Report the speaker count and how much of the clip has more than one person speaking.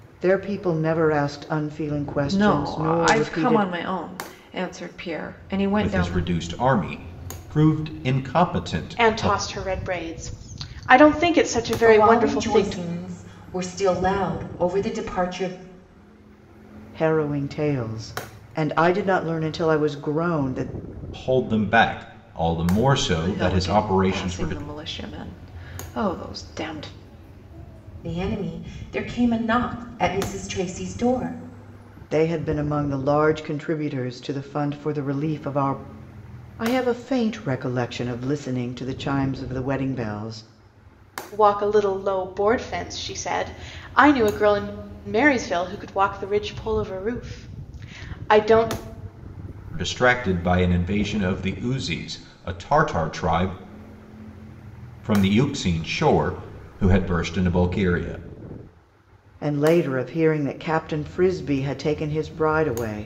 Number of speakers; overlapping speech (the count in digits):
5, about 8%